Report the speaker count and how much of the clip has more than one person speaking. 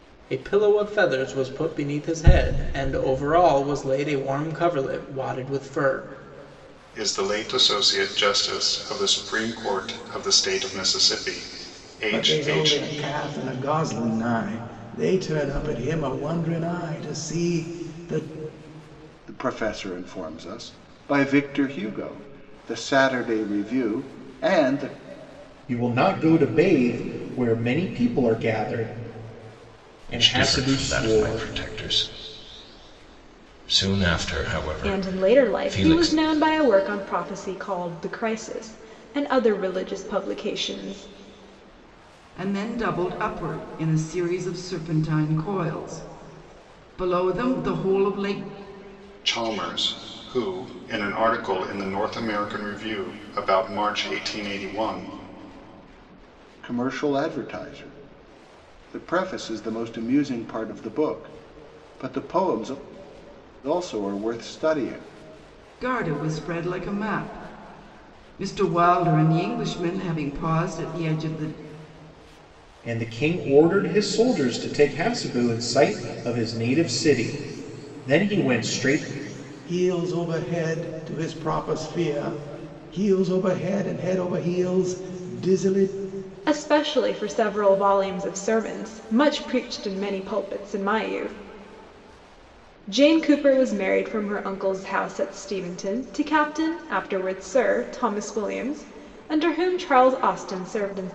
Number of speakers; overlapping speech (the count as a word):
eight, about 3%